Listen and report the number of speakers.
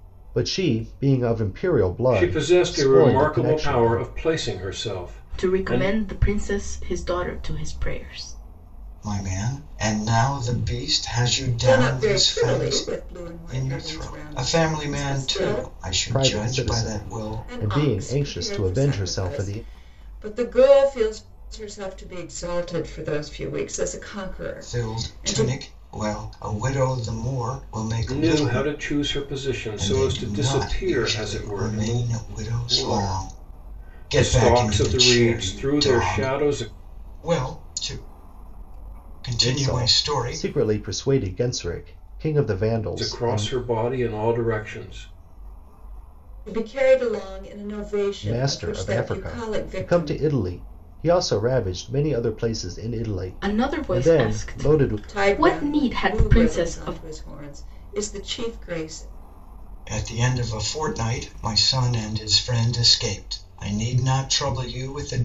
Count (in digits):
5